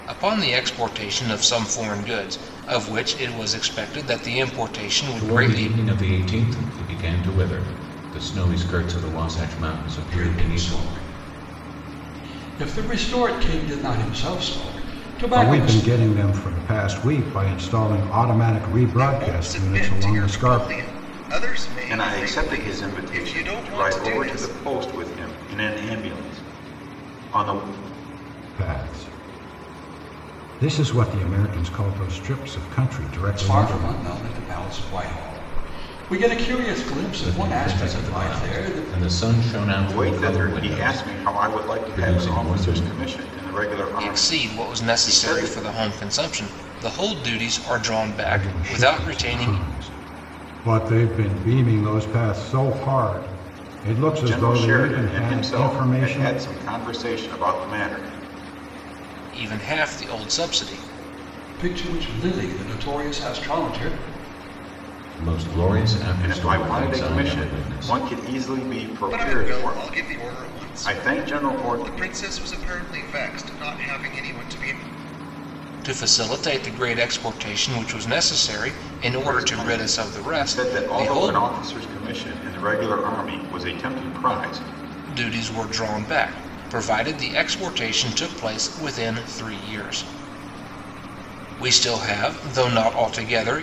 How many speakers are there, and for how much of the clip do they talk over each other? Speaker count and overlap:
six, about 26%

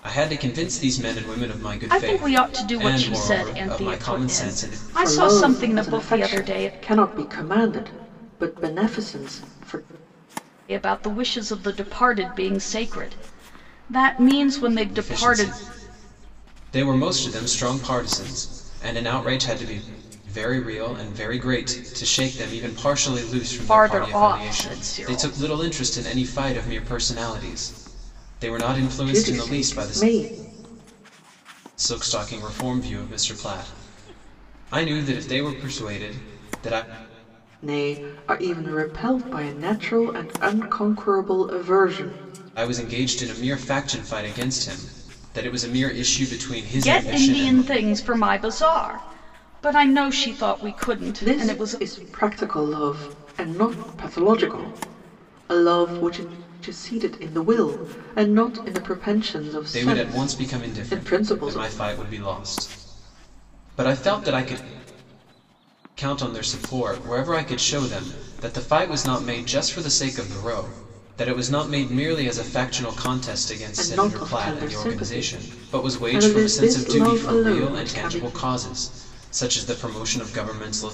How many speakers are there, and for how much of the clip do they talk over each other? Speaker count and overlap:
three, about 20%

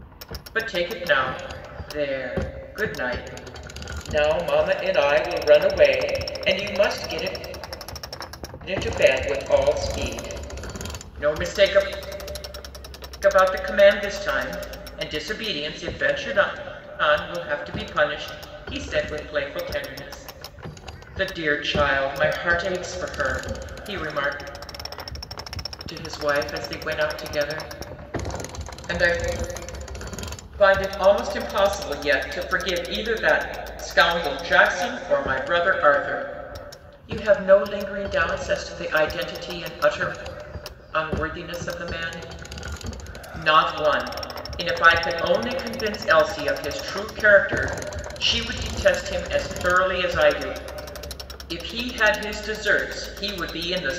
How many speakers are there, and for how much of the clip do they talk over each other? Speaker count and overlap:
one, no overlap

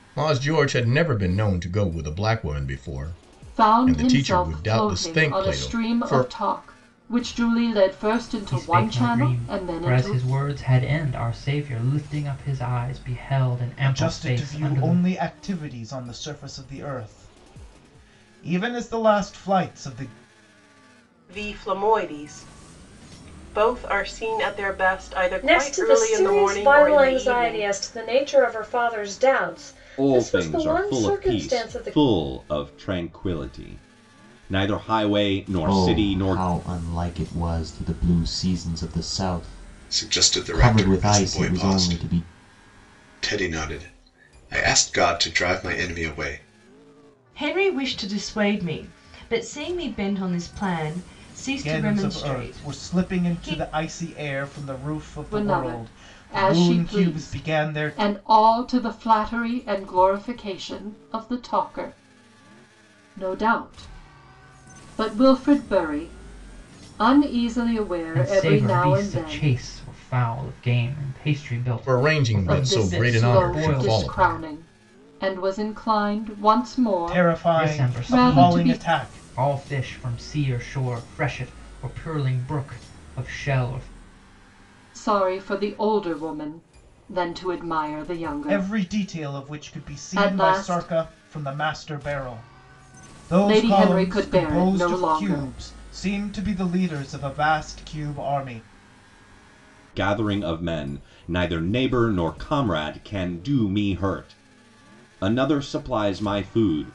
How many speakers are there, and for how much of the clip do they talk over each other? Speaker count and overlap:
ten, about 27%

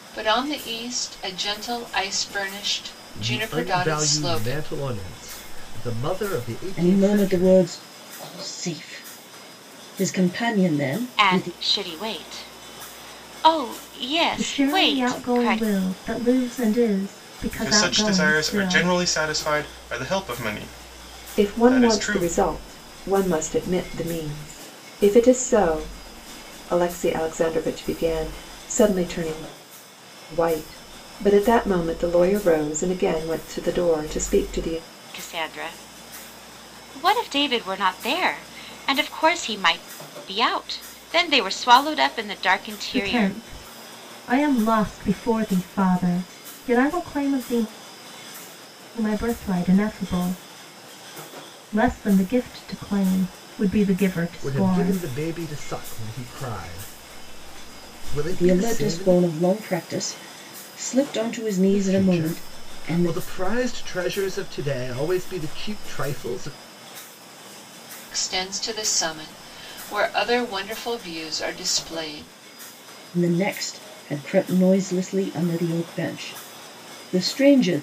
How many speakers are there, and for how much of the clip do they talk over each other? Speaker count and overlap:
seven, about 13%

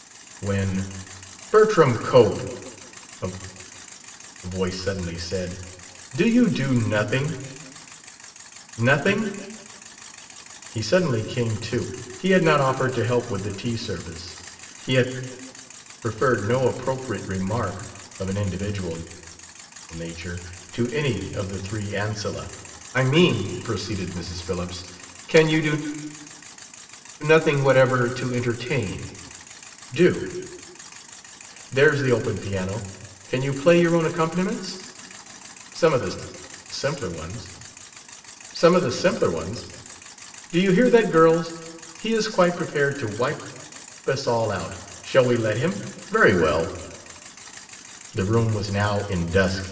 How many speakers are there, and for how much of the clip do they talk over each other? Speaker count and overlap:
one, no overlap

